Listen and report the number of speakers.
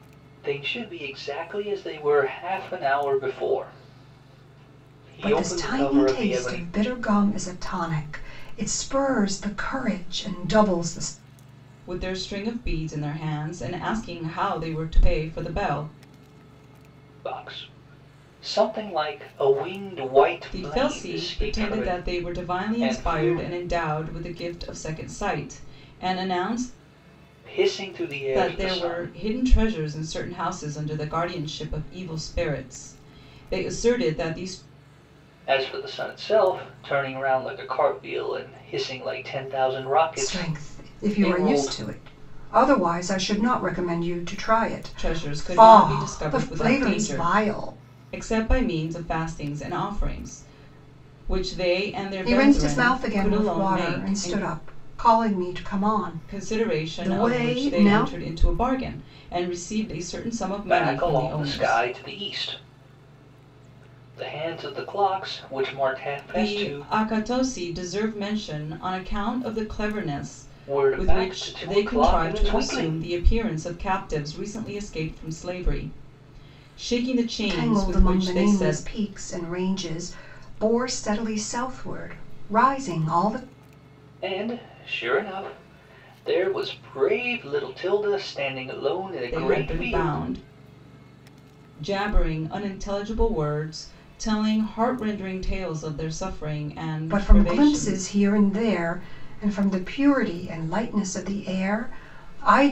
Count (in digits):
3